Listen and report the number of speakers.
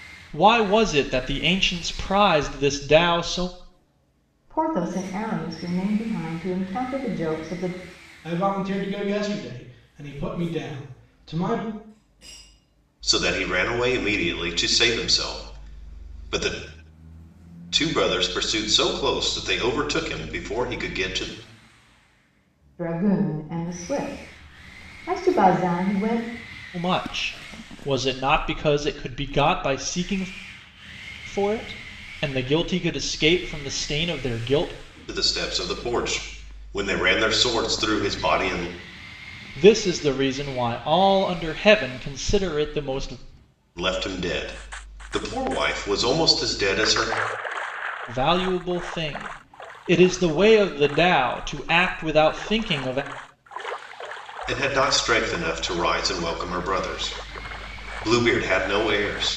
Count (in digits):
4